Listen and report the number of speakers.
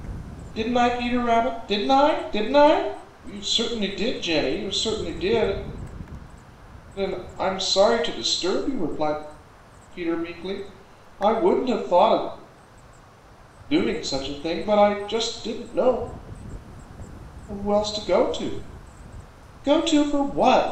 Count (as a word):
one